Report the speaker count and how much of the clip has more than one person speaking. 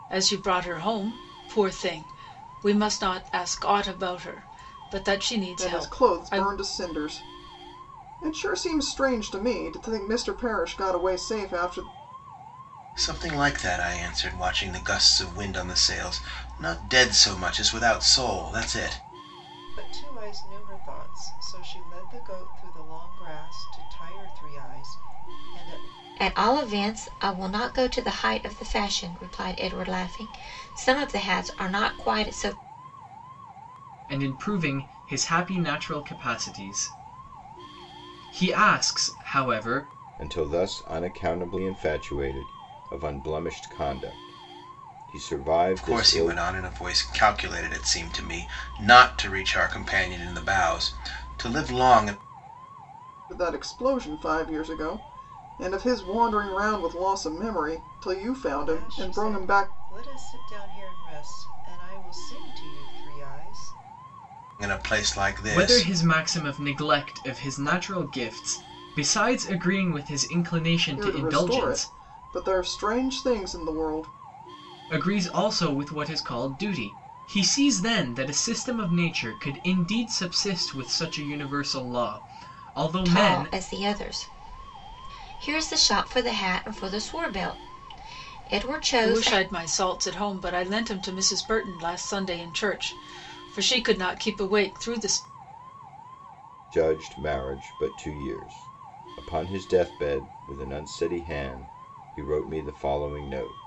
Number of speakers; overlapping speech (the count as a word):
seven, about 5%